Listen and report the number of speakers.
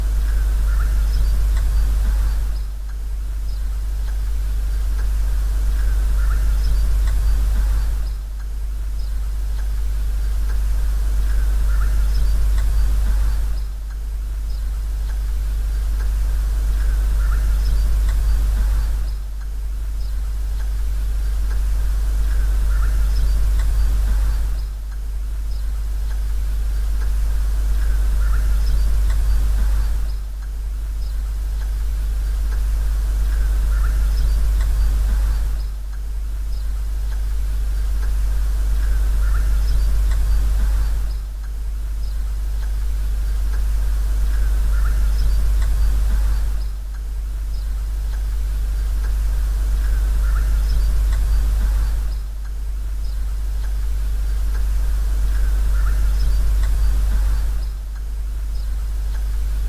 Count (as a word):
zero